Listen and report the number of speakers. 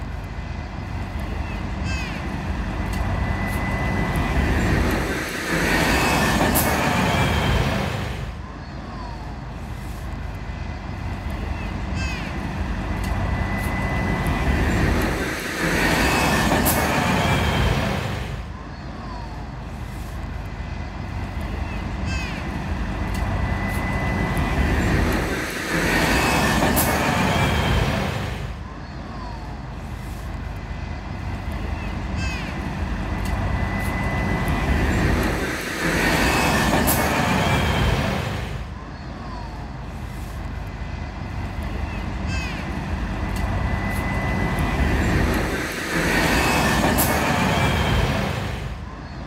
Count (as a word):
zero